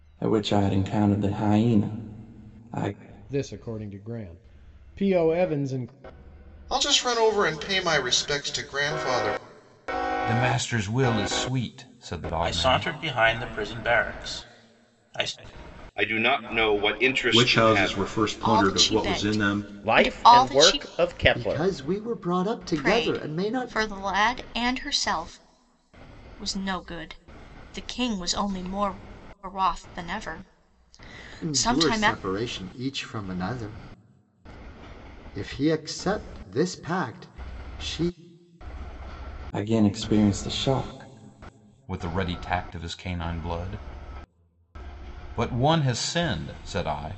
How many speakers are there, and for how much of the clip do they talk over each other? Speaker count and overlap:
ten, about 12%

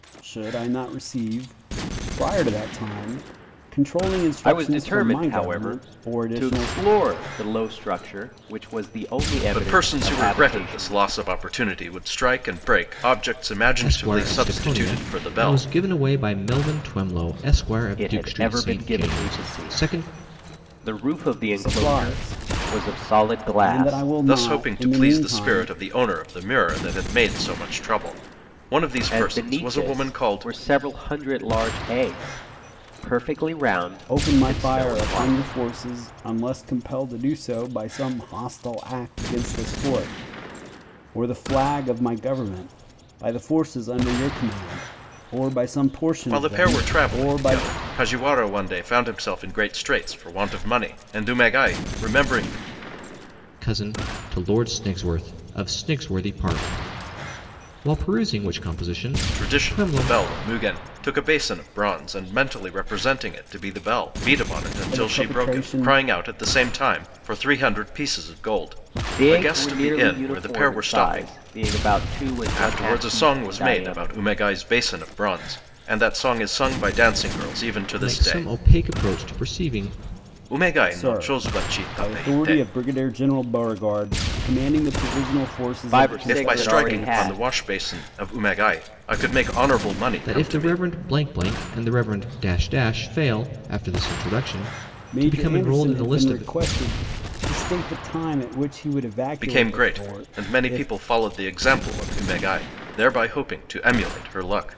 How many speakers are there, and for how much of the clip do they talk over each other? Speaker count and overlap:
four, about 29%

